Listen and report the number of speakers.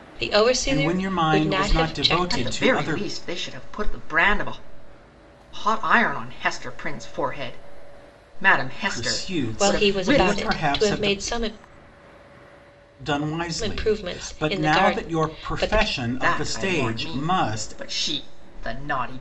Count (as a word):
three